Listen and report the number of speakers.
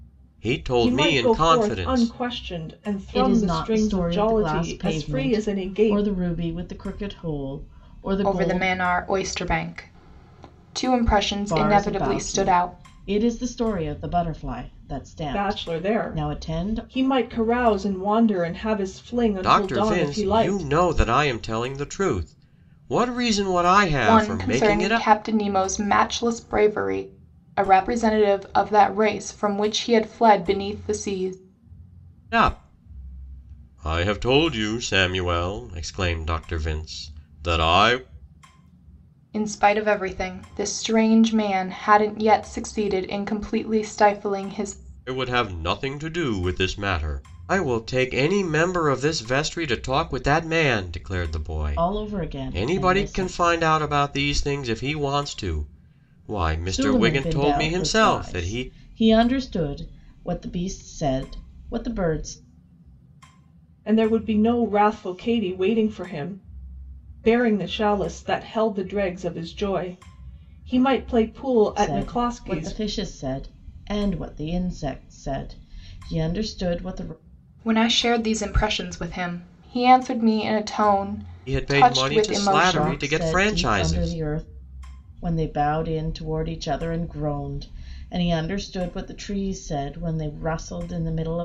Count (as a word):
four